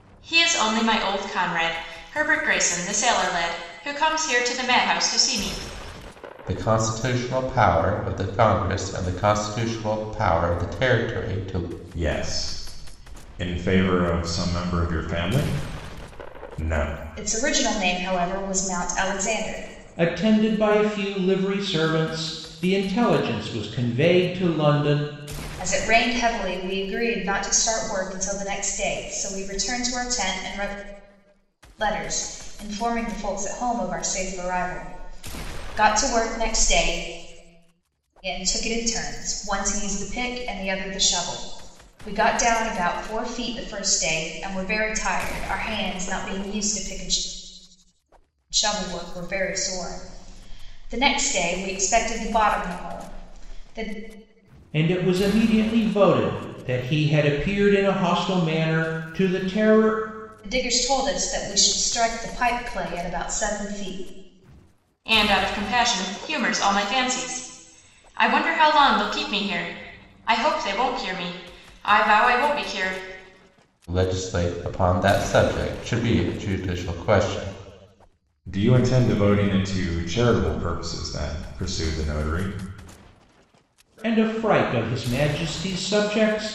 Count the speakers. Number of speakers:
5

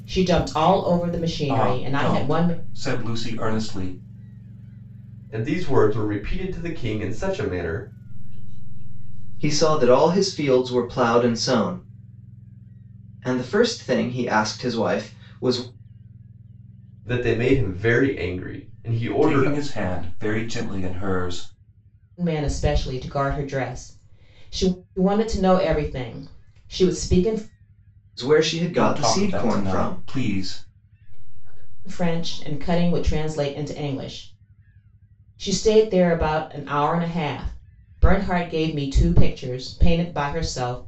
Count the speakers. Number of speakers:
5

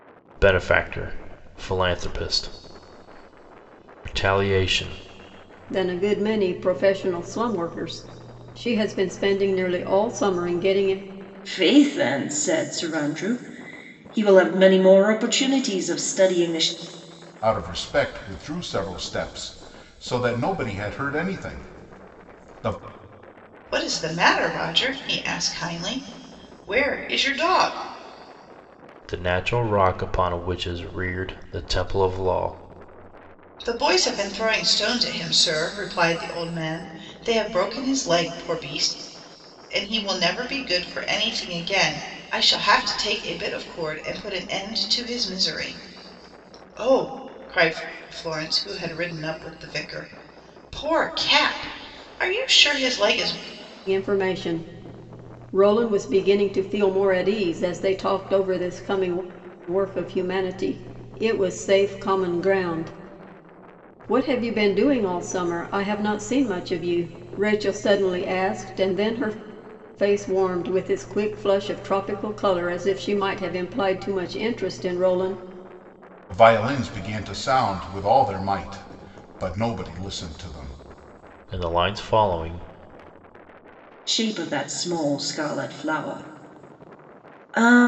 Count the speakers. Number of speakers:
5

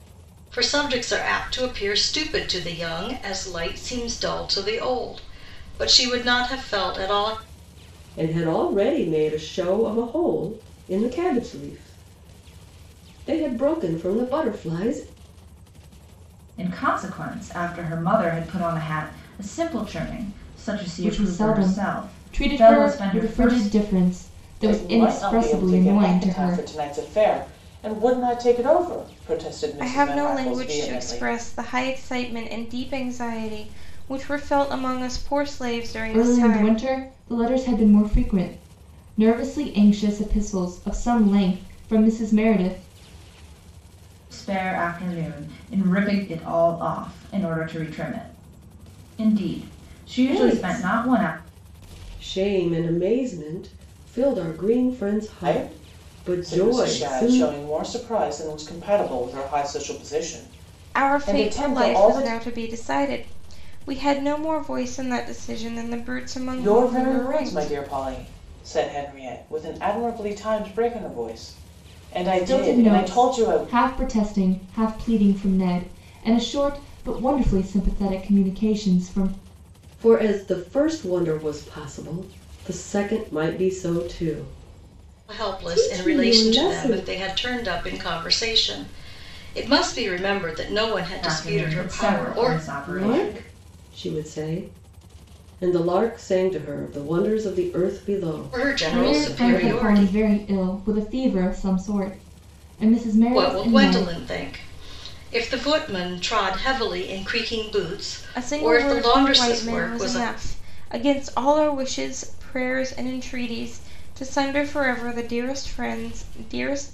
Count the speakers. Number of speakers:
6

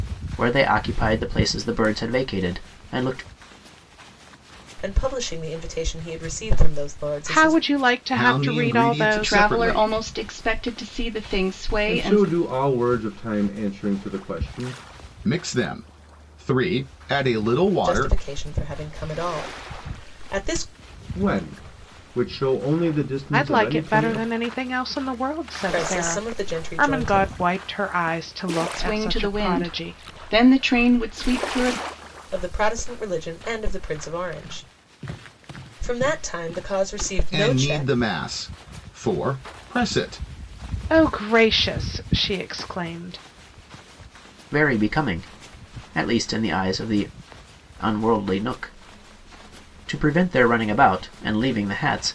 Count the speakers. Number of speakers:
6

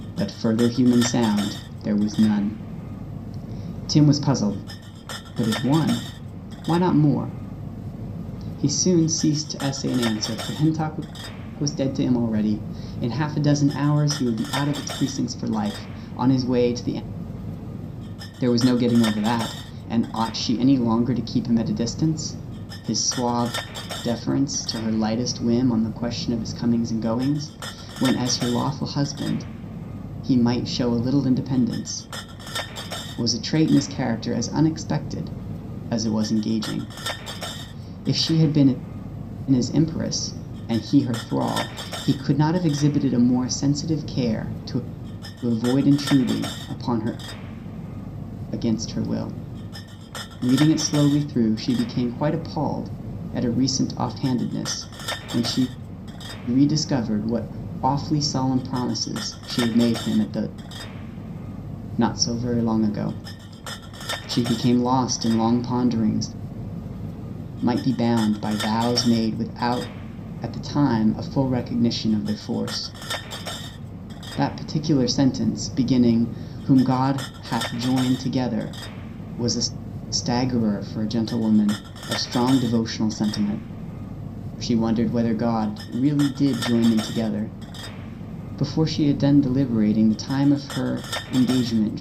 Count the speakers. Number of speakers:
1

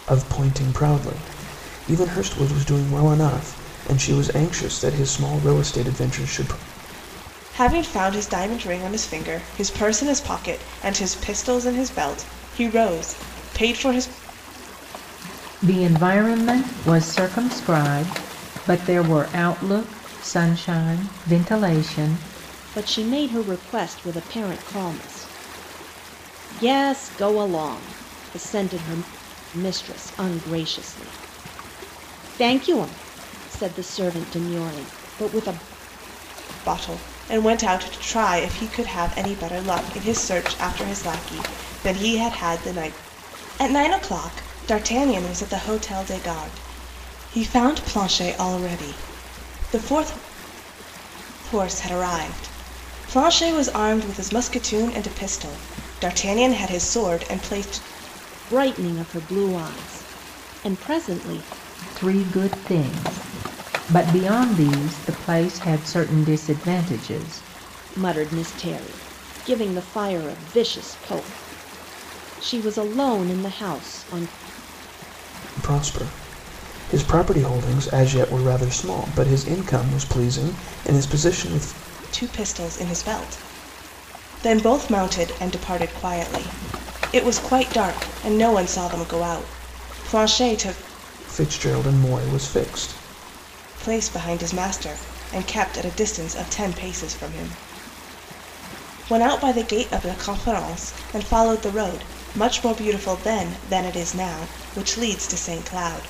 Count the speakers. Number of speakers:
4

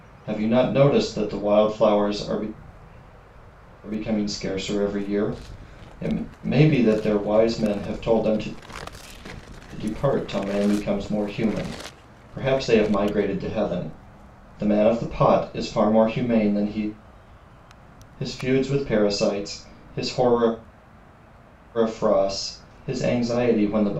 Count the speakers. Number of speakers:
1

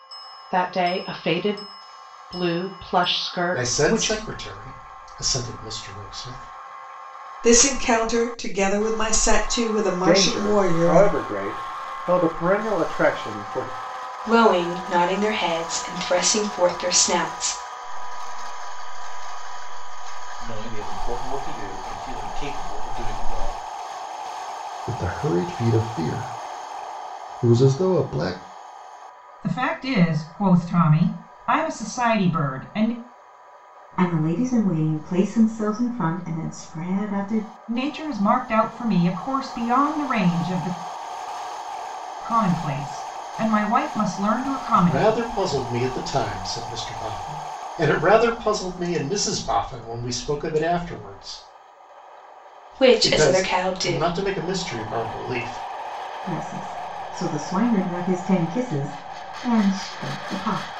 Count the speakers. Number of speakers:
10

